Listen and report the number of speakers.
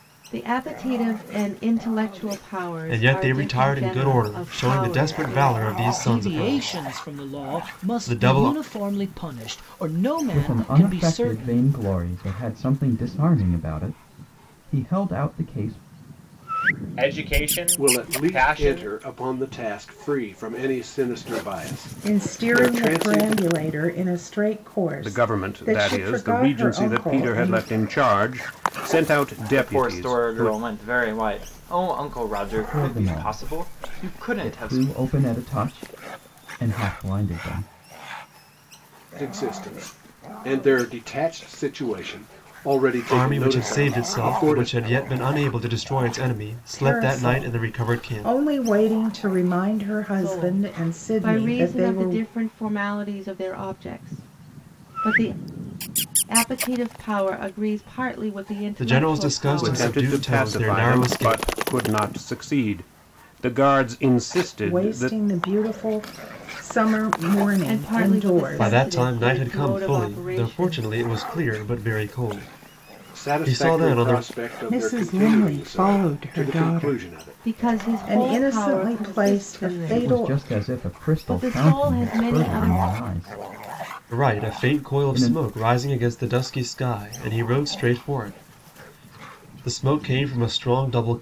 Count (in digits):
9